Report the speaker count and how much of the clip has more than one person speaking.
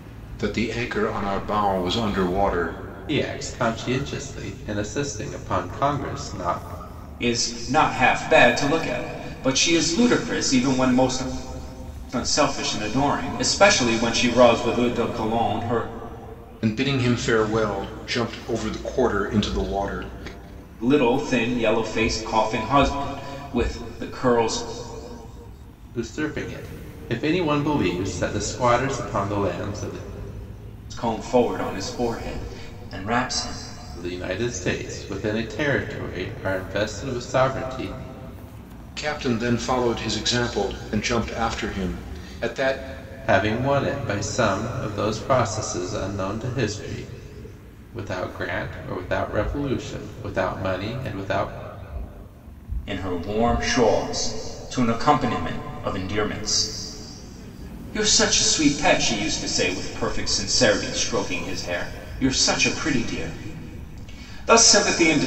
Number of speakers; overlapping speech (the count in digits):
3, no overlap